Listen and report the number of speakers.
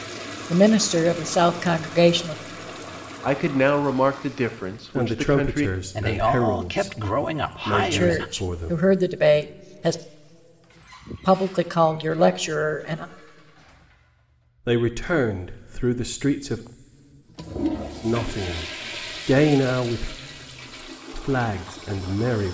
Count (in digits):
4